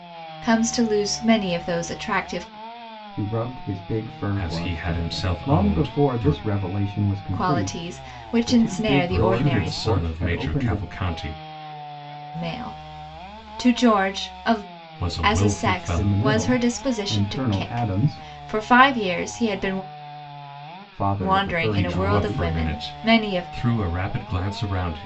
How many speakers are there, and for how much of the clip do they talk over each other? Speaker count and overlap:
3, about 41%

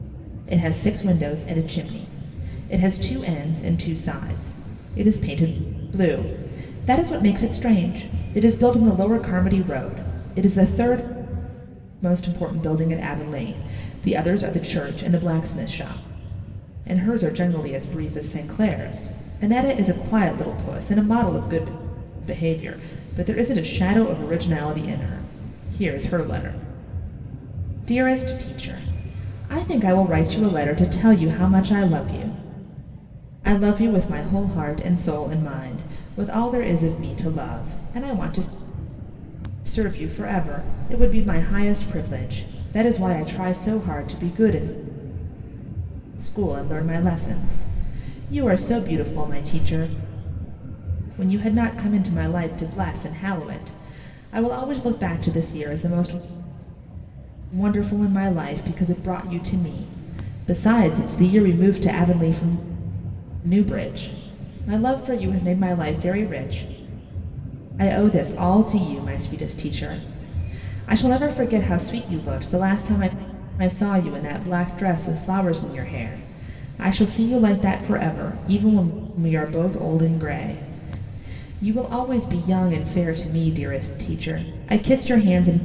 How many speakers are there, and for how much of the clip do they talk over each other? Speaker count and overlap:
1, no overlap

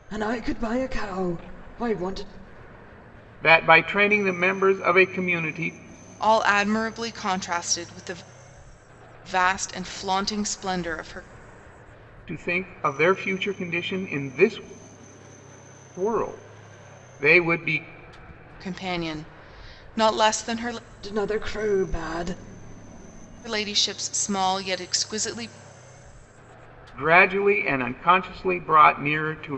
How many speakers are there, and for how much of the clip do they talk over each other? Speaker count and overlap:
3, no overlap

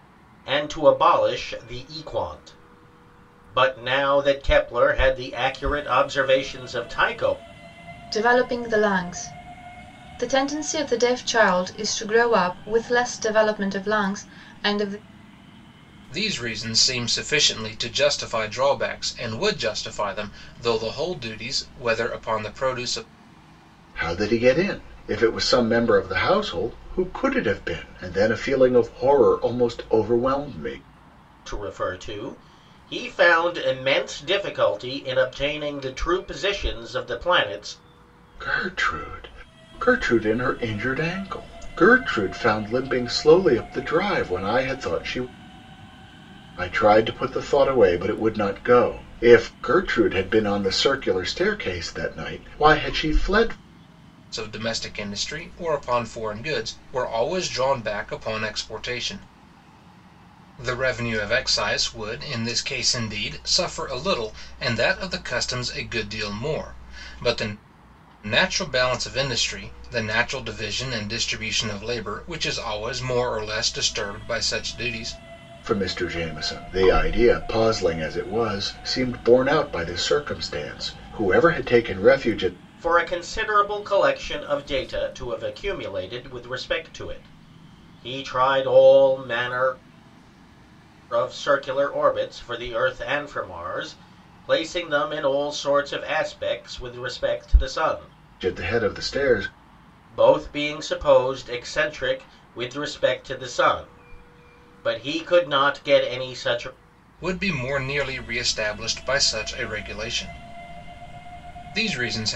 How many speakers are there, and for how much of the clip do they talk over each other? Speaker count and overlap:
4, no overlap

